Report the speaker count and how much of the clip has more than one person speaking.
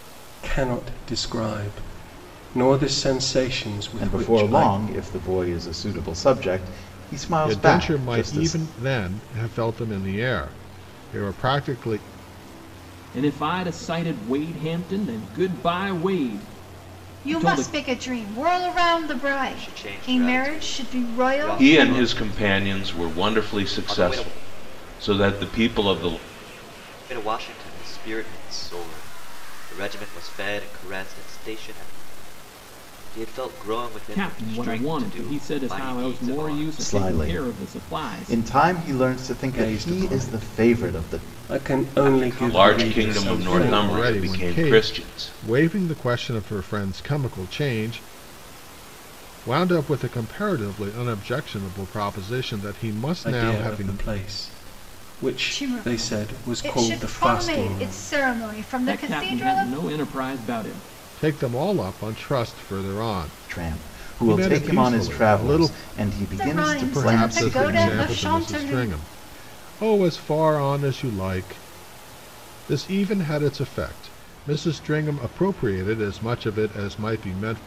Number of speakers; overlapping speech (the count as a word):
seven, about 34%